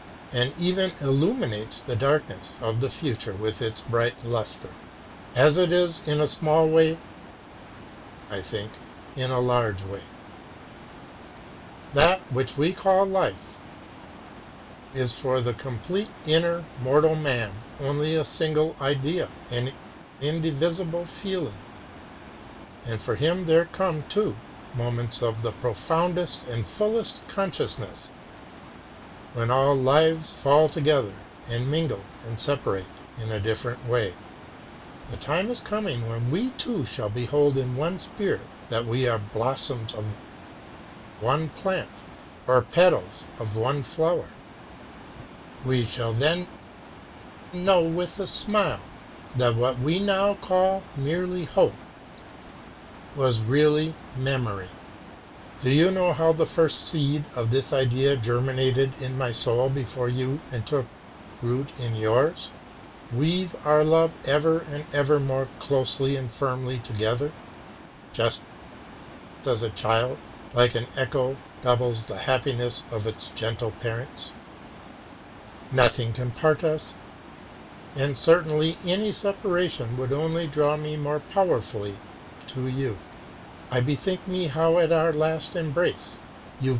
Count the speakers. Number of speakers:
1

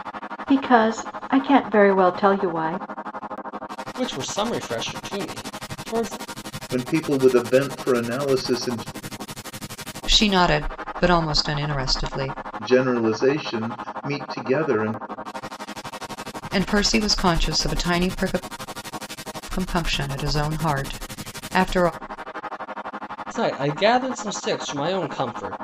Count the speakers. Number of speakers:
4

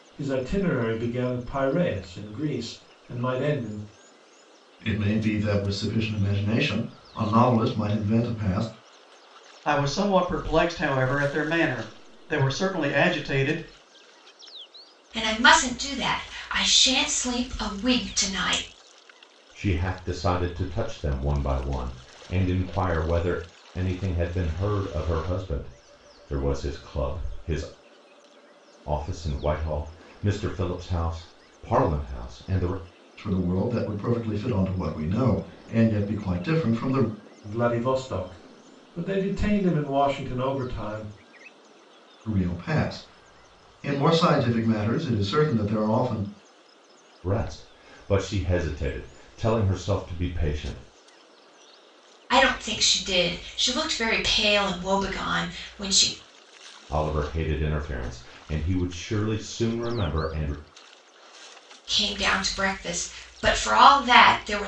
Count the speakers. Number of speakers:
5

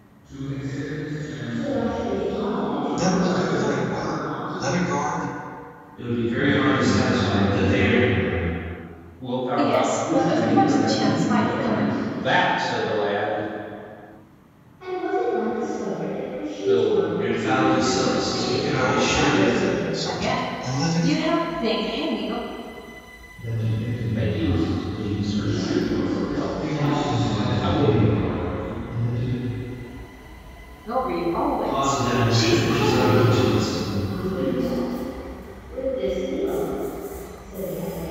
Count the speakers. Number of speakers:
9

